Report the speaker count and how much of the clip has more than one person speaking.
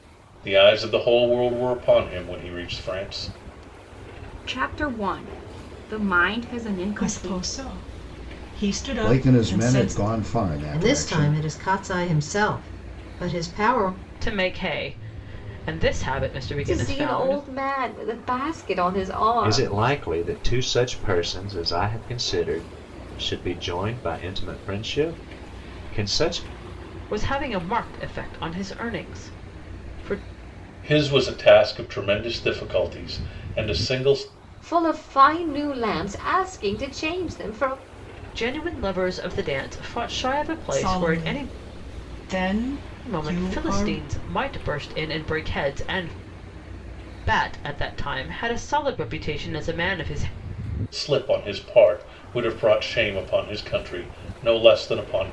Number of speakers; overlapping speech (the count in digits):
8, about 9%